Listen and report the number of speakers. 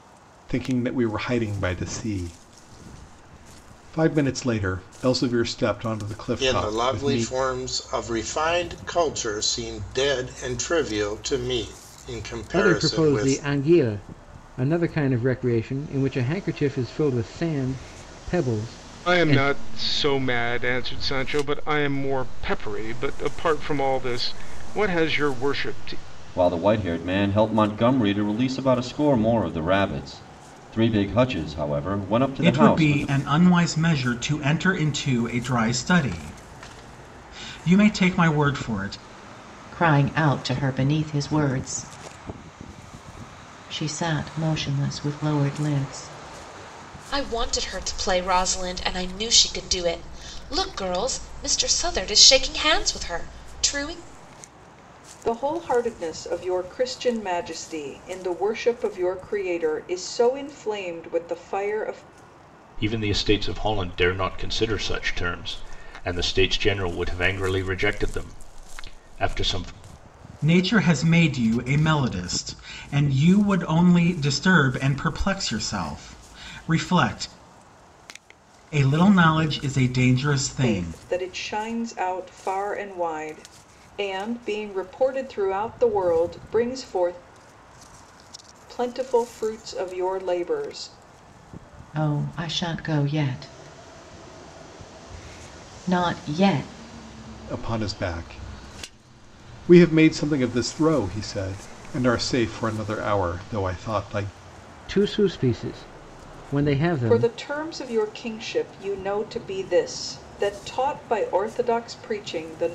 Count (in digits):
10